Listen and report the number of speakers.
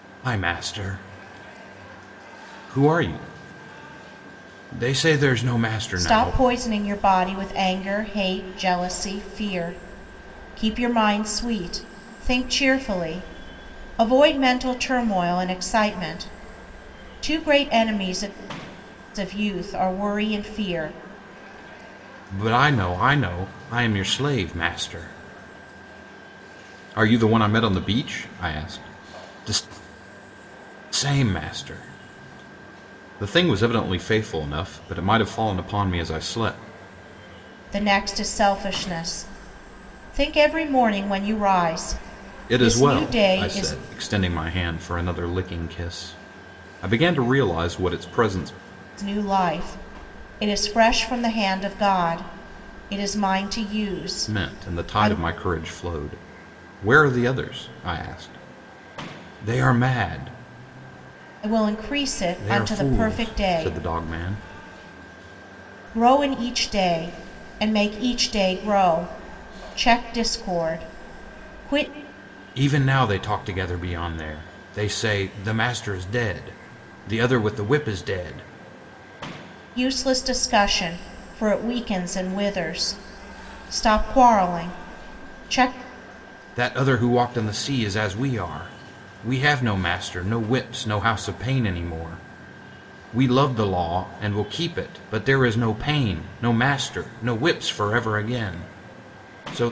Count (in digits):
2